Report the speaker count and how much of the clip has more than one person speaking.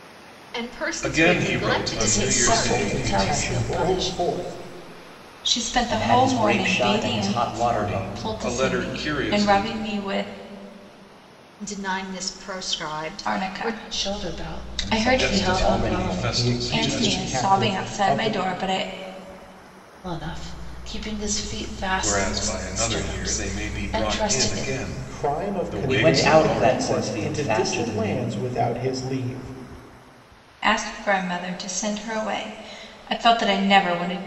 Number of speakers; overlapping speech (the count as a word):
six, about 51%